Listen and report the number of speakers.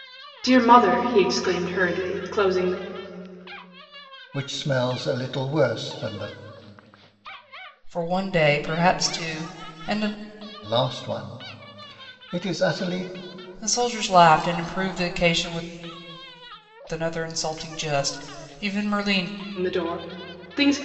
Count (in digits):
3